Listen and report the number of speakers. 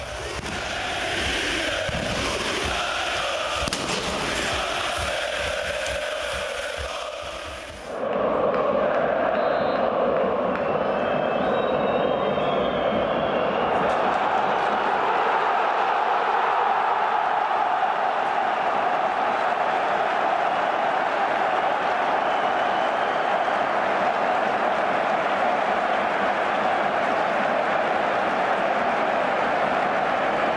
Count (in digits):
0